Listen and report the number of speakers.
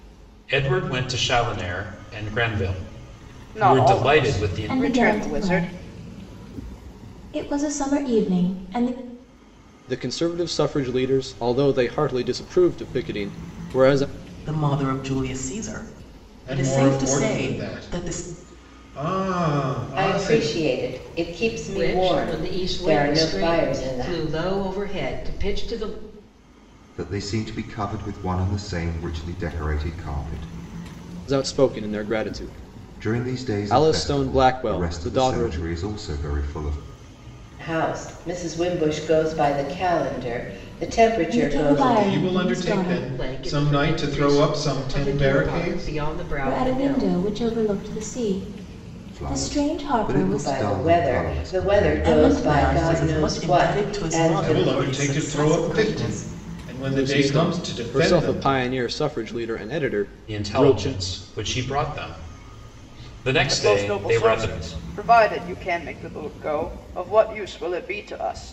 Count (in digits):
9